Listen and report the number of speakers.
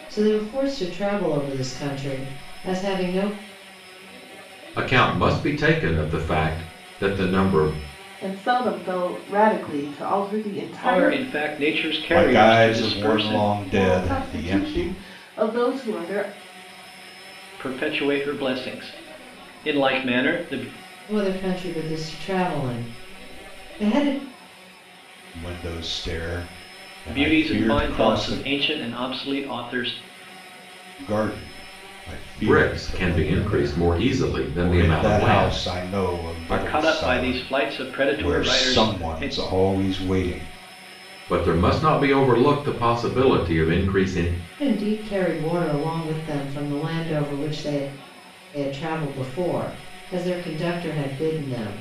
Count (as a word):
five